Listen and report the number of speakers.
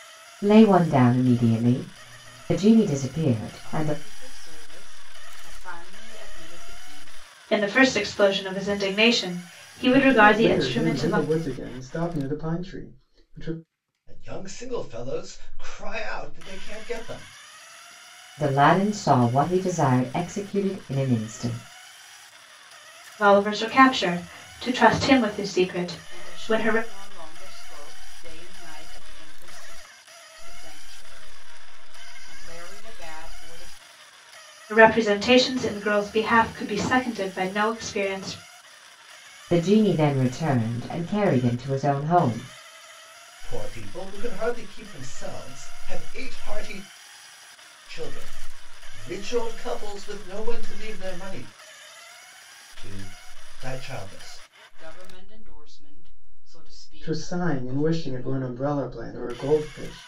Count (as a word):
five